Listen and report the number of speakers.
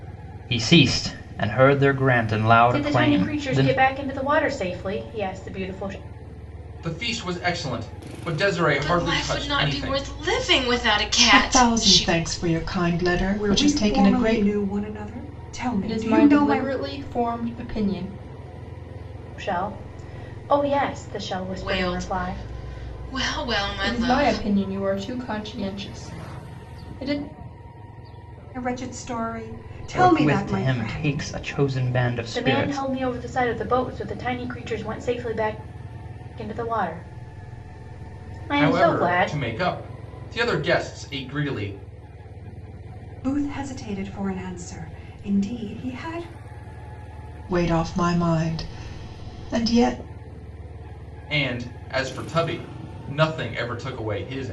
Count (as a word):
seven